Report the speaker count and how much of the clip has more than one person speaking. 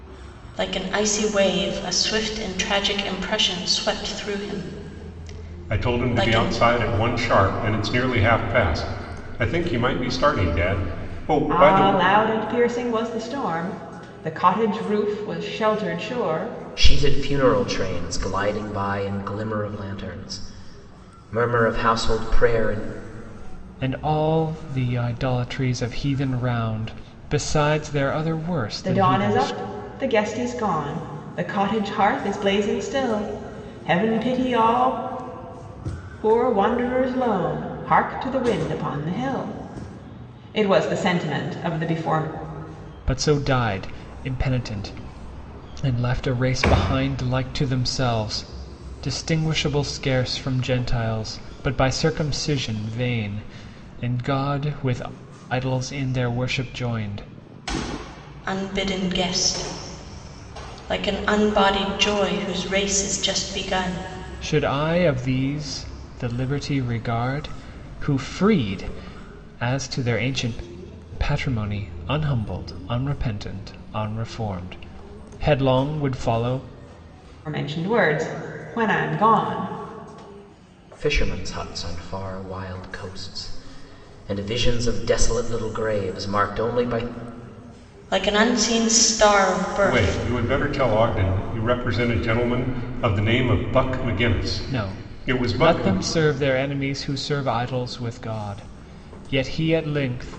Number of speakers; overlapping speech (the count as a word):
five, about 4%